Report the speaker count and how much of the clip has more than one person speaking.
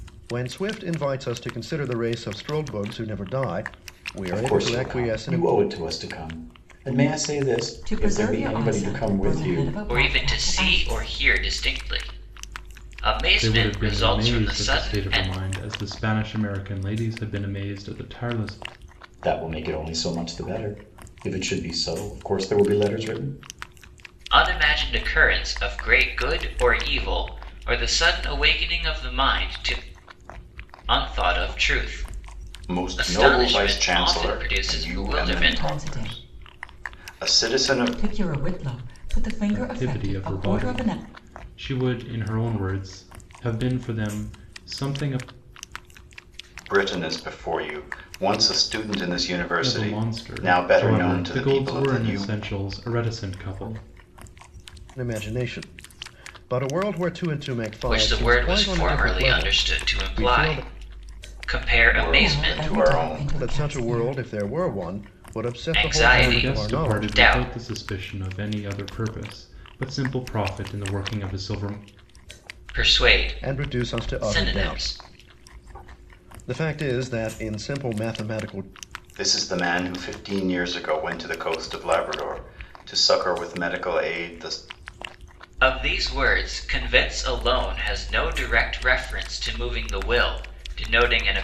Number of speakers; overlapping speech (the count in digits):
5, about 27%